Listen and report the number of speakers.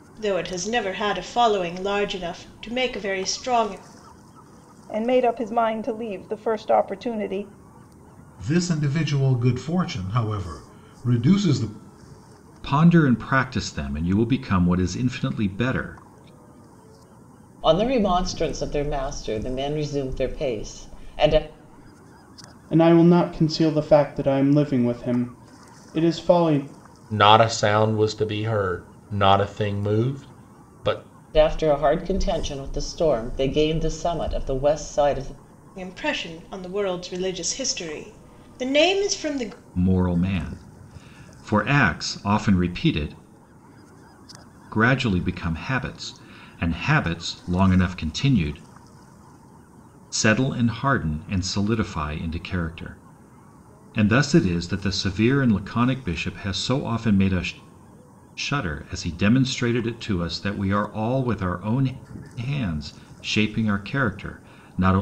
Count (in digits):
7